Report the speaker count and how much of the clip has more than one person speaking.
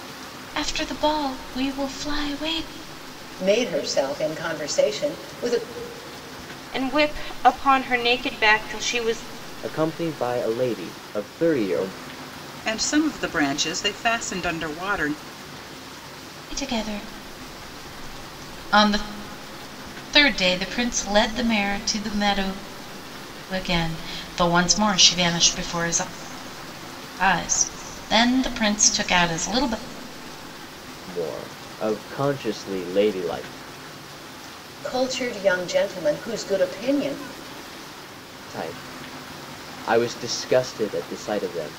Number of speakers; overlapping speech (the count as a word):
five, no overlap